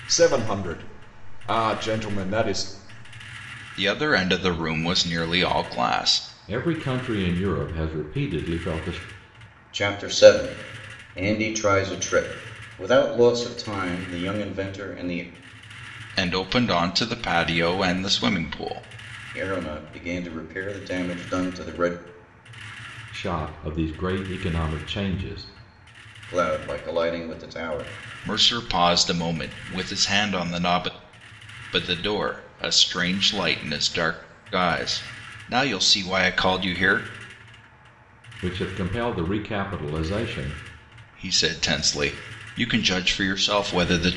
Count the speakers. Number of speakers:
four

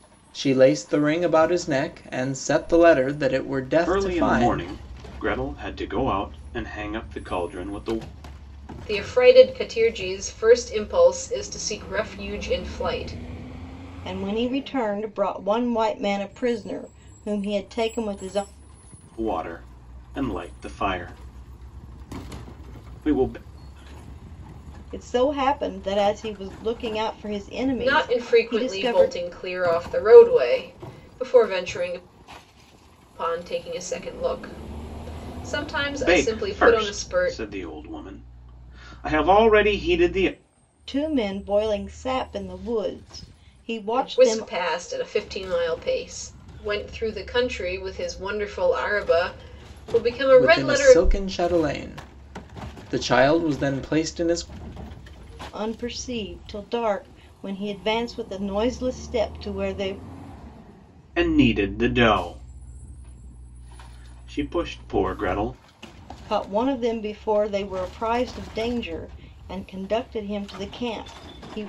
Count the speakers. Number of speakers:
four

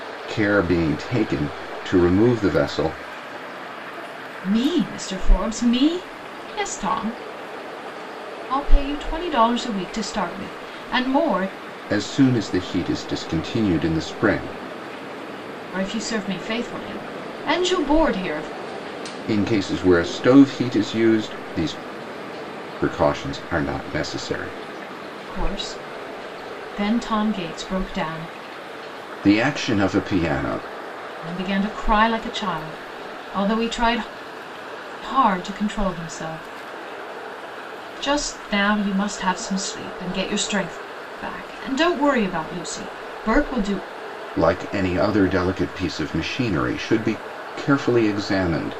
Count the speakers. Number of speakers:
two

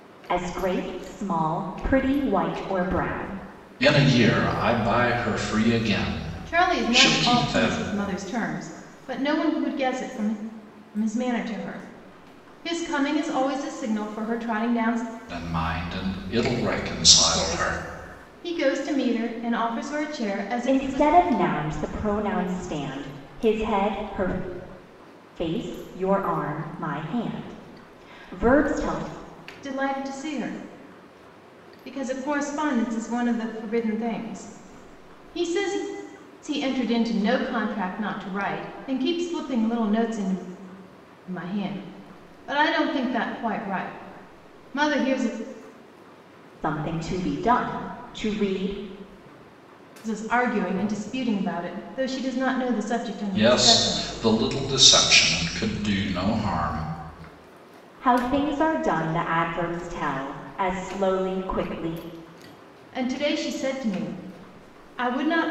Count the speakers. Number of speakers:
three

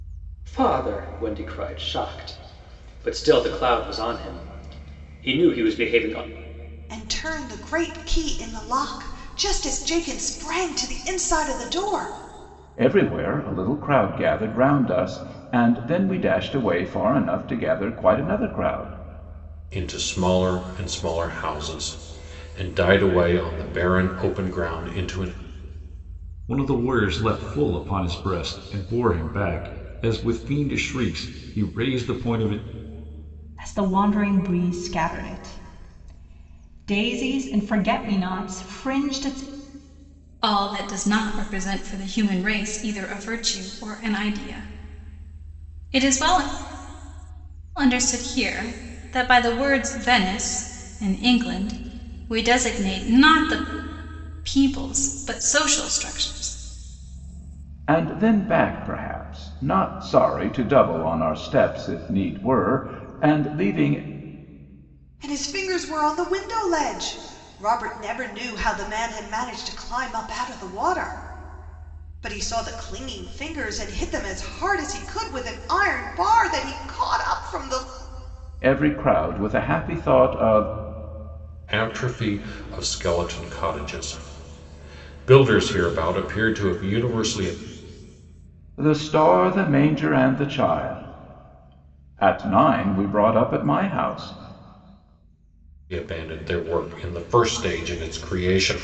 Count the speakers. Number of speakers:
seven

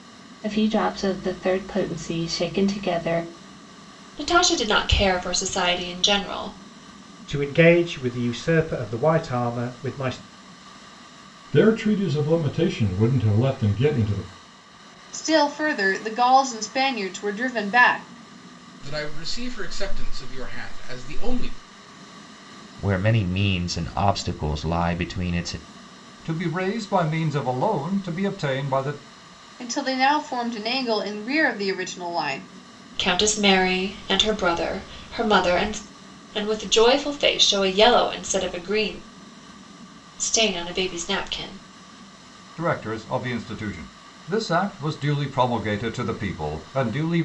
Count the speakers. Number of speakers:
eight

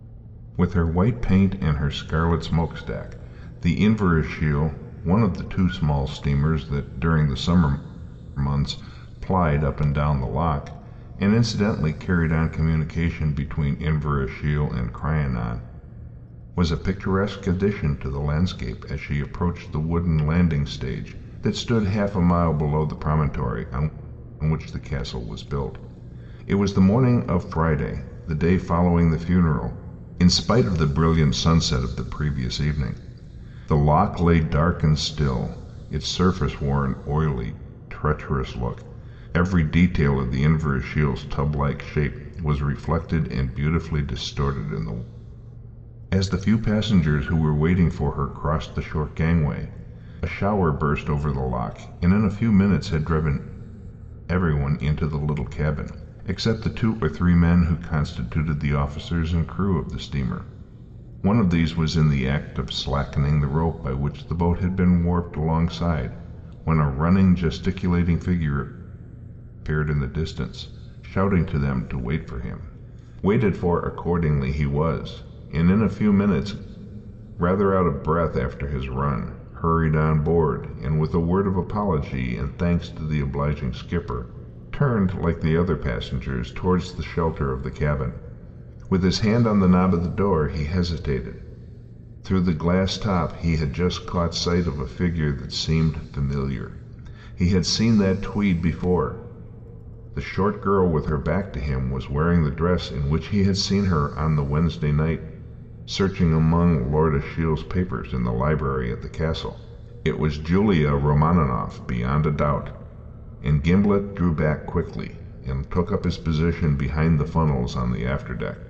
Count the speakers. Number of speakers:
one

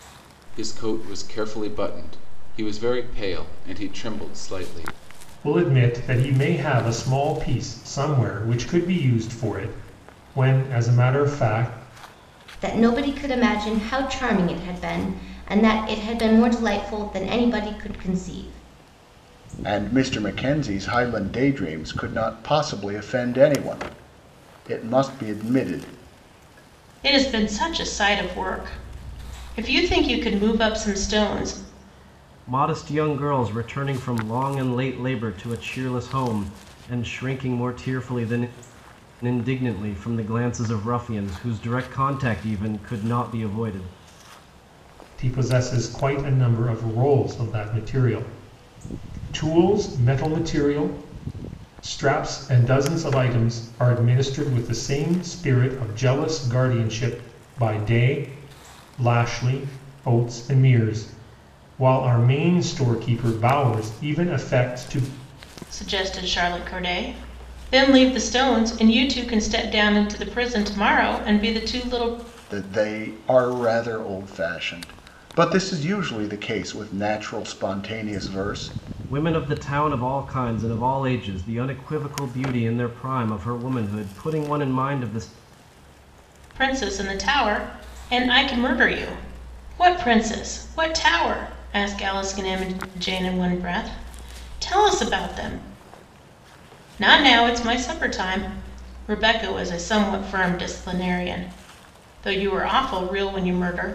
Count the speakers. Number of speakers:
six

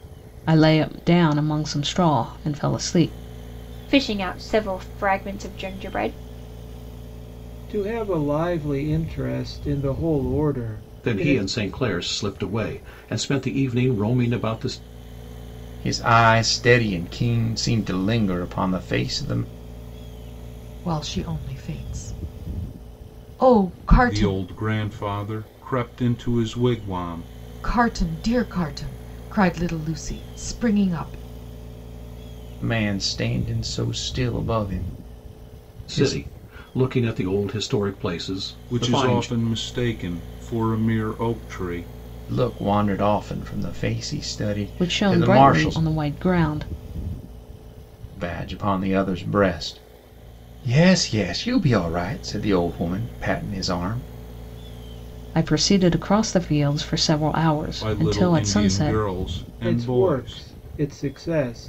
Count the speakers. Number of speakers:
seven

